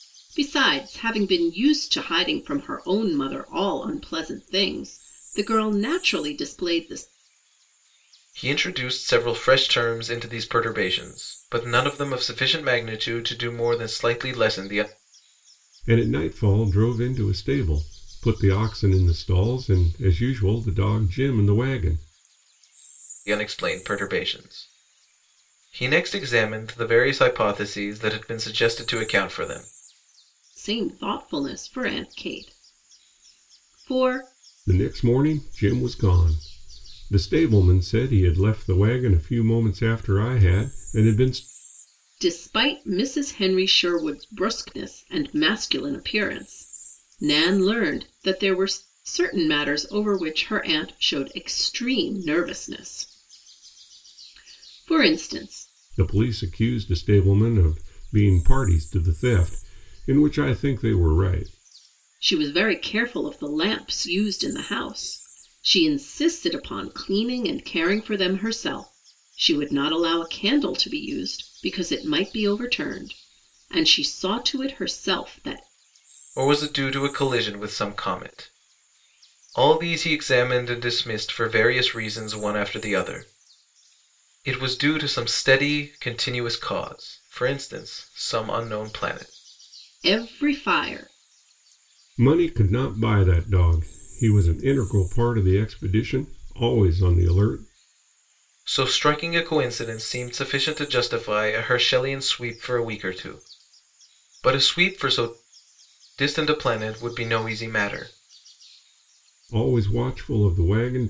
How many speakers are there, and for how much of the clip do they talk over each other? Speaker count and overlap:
3, no overlap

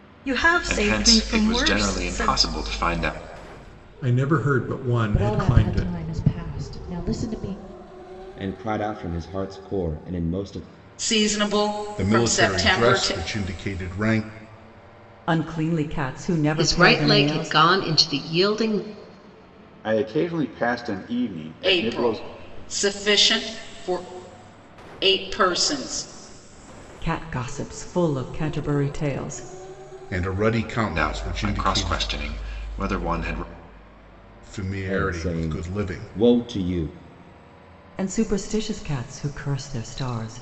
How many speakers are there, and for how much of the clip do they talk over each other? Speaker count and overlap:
10, about 20%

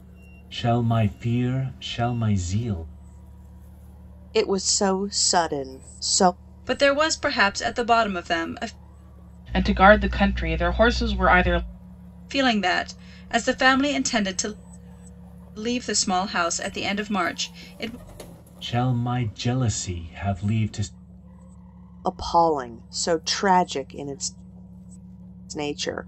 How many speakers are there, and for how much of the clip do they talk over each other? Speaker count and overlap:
4, no overlap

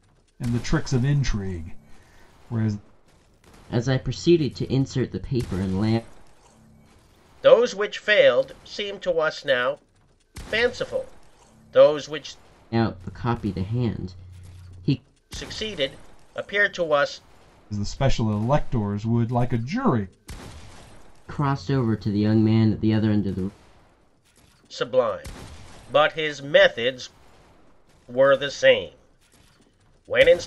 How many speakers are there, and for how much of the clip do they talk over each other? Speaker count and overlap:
3, no overlap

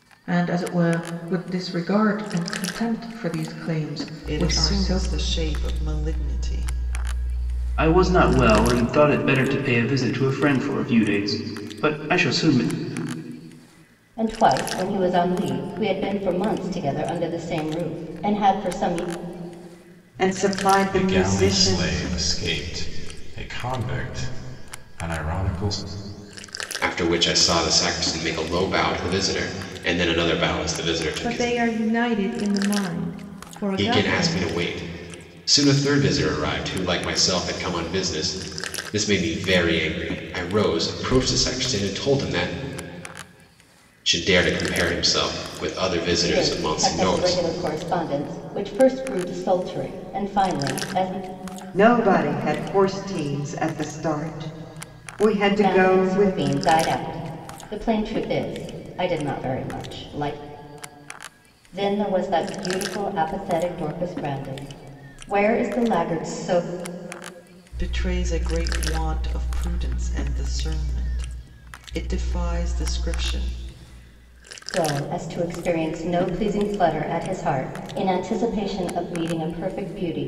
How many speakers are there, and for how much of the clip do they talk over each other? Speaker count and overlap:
8, about 8%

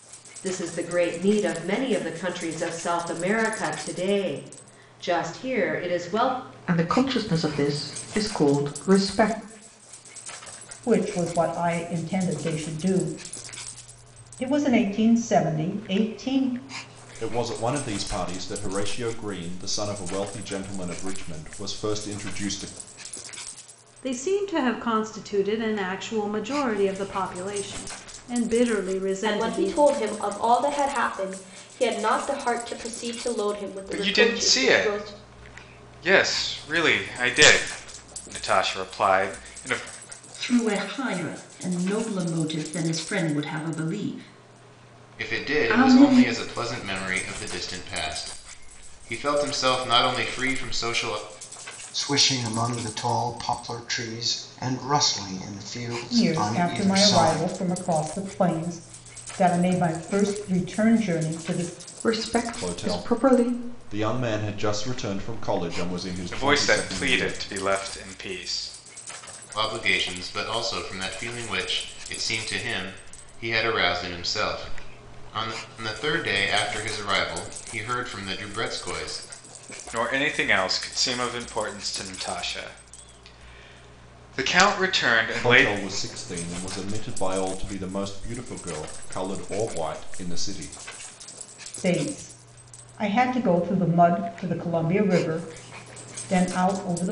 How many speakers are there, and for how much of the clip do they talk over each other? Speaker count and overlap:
10, about 7%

